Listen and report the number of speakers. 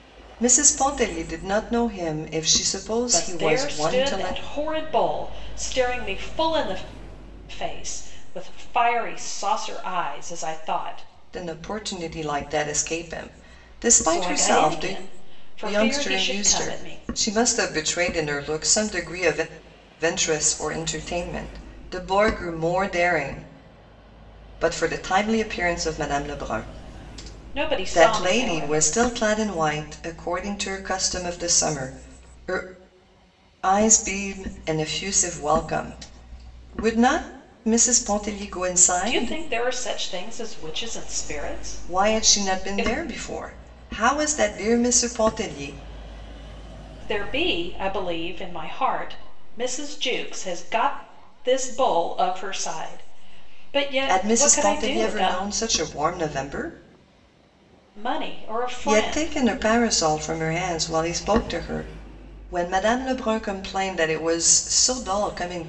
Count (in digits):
2